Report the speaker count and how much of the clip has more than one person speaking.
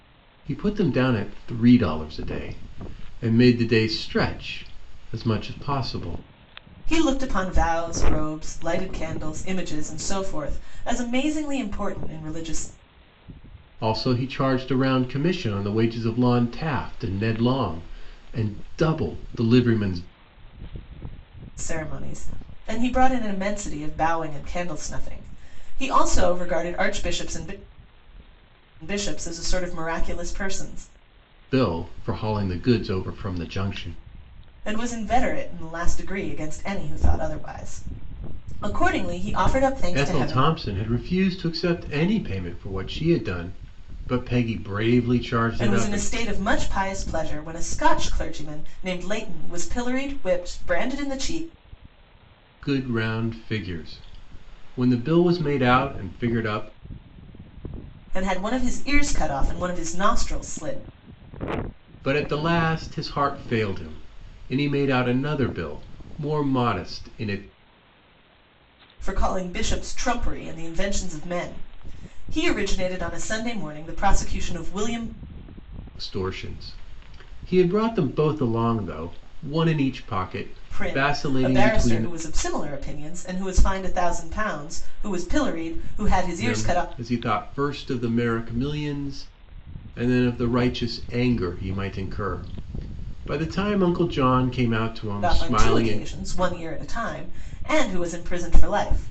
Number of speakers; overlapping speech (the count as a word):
two, about 4%